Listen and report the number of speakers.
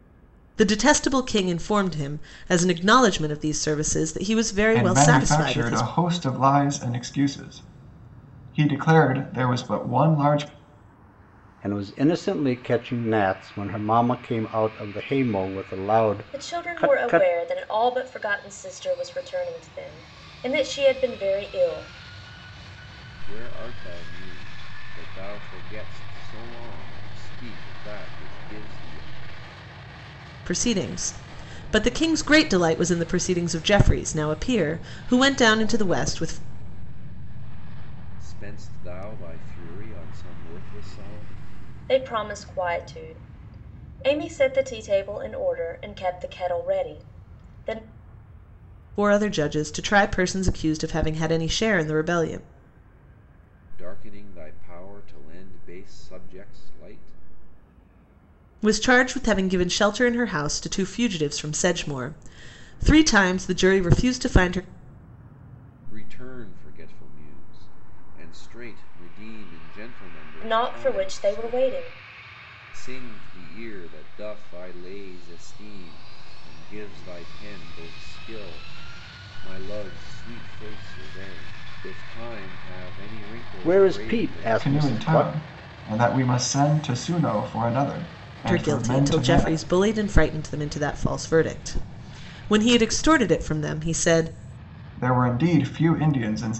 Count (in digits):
5